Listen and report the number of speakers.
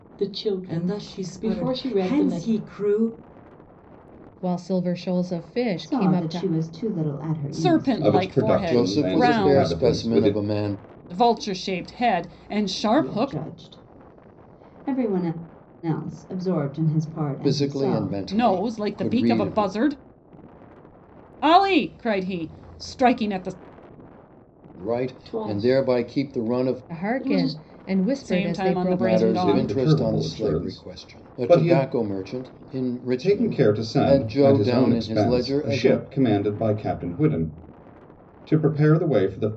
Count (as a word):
seven